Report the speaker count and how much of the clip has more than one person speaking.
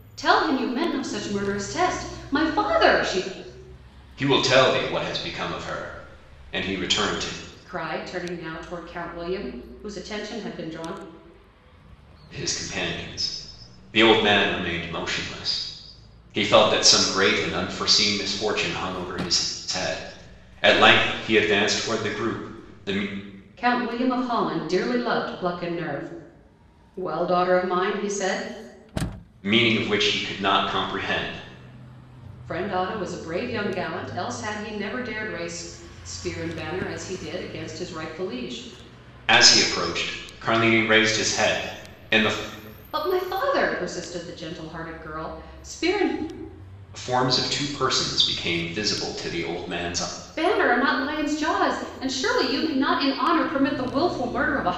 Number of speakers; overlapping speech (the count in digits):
2, no overlap